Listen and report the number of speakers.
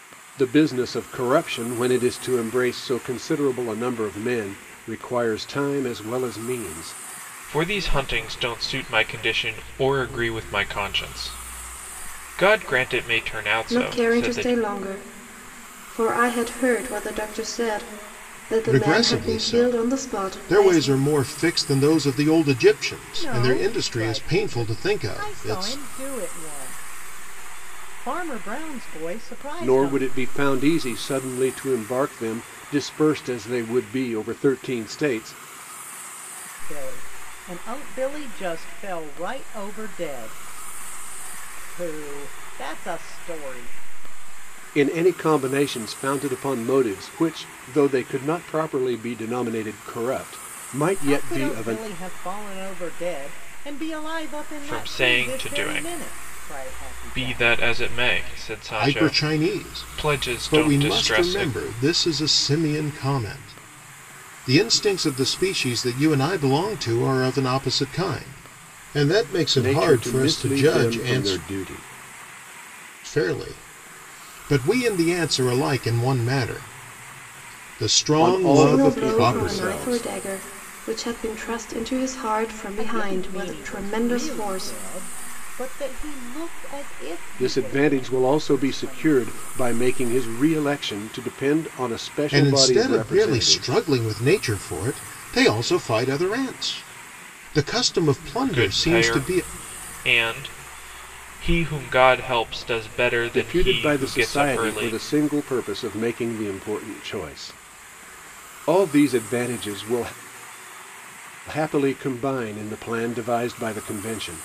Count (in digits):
5